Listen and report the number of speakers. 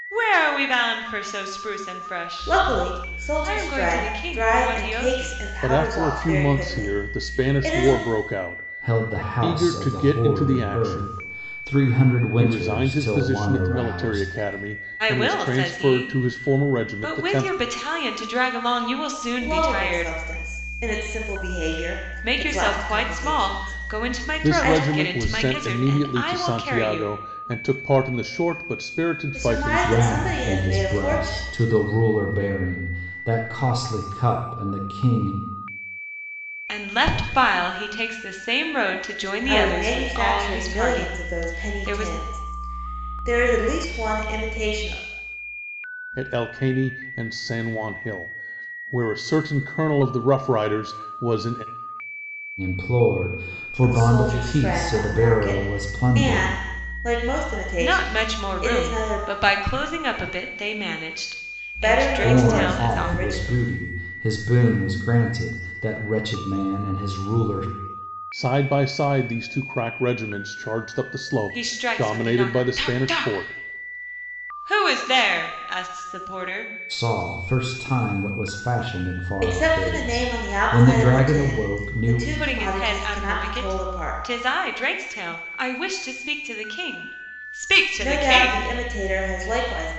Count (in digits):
4